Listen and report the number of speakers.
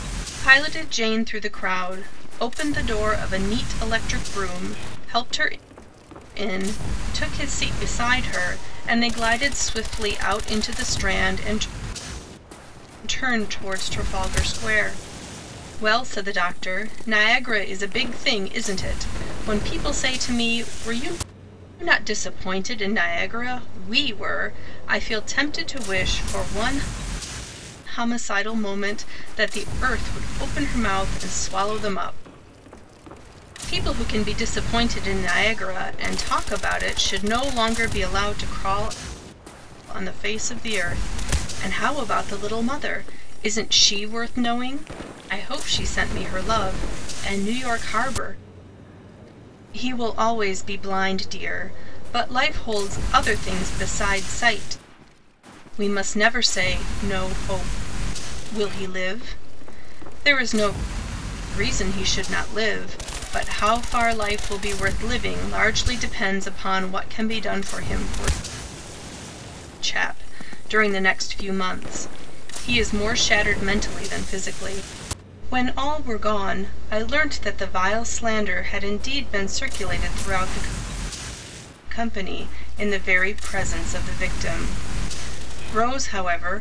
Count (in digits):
1